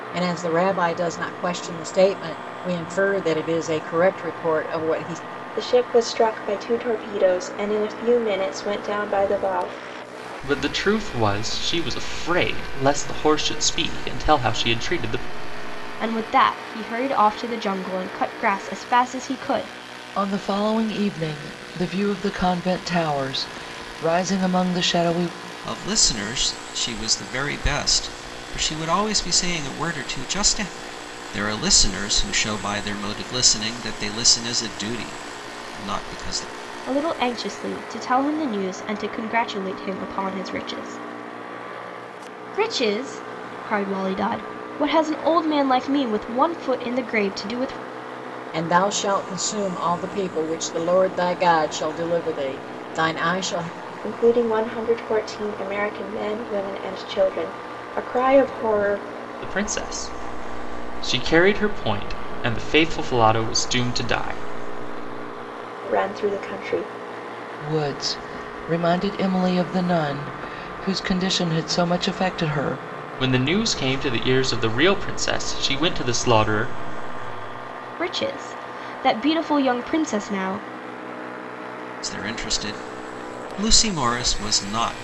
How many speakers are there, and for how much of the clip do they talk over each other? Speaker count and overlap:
6, no overlap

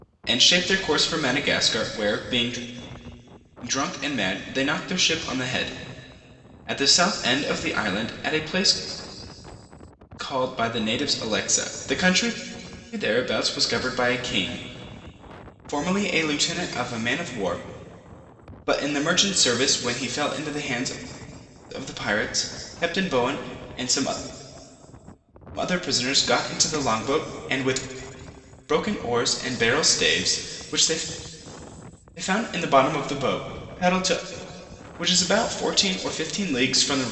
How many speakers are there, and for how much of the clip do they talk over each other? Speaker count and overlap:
1, no overlap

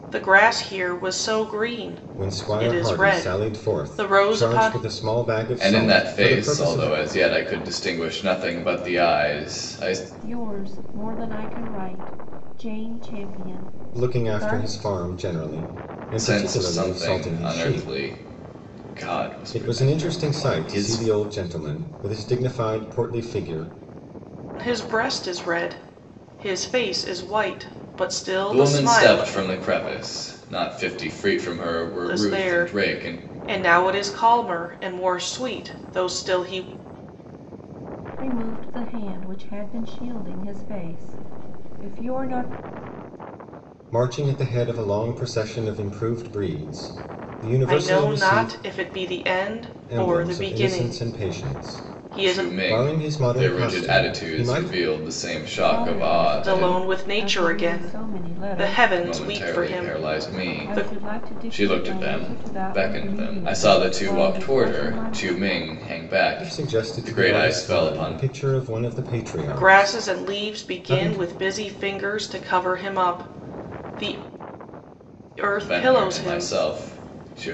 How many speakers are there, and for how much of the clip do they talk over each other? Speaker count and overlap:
4, about 39%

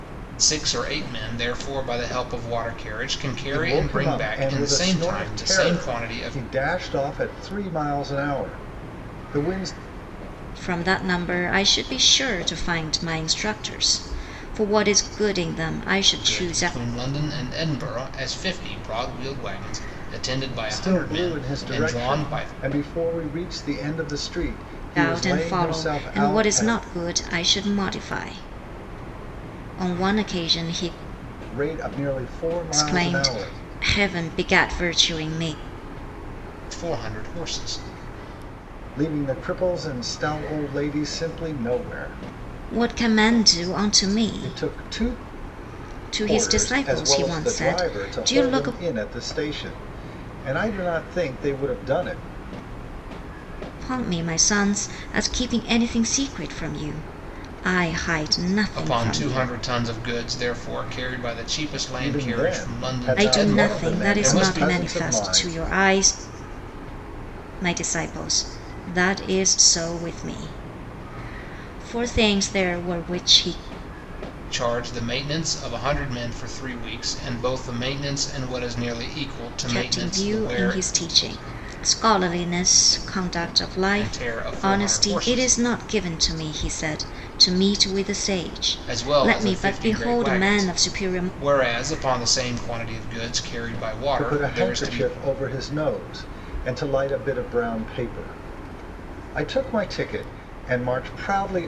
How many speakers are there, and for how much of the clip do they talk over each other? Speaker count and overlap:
3, about 24%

